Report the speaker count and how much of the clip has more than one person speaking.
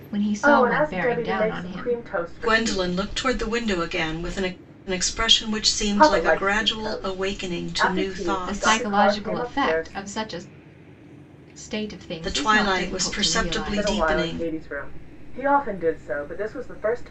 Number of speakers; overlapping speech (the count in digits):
3, about 47%